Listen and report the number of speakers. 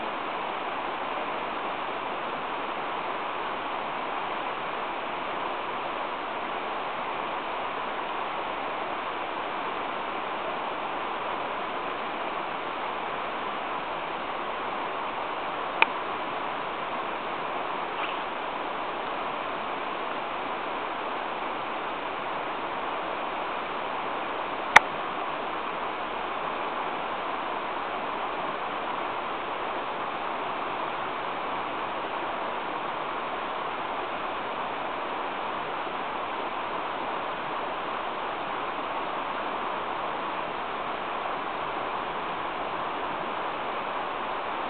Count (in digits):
0